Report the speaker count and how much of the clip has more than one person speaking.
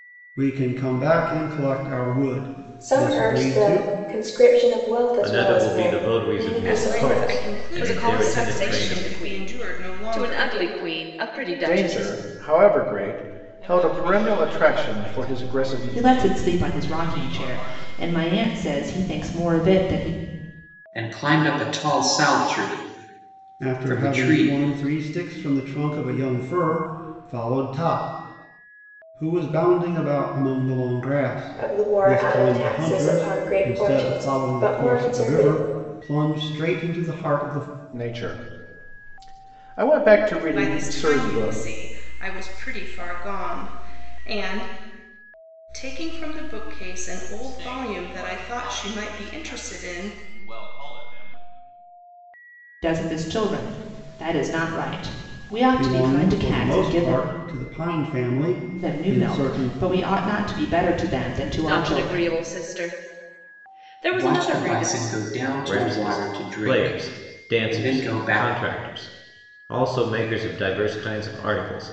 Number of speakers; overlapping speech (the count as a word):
nine, about 39%